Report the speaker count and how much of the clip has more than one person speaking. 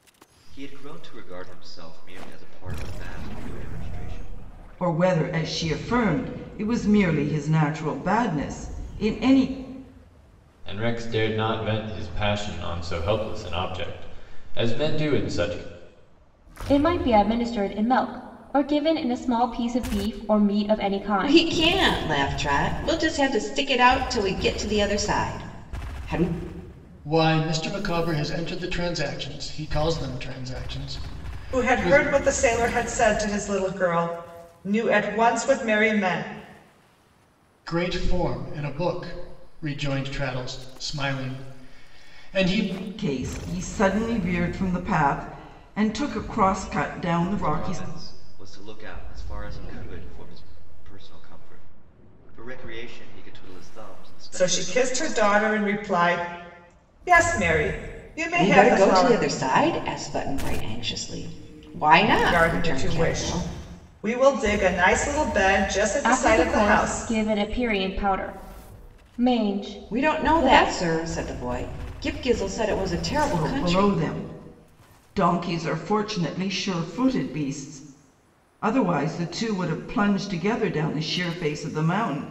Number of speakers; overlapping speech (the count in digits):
7, about 9%